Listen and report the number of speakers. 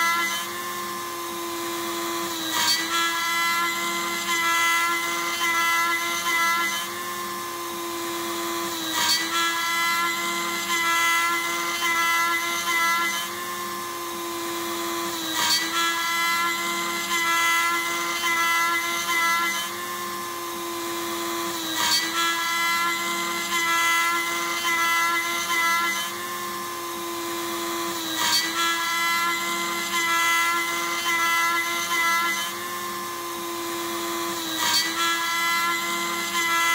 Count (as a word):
zero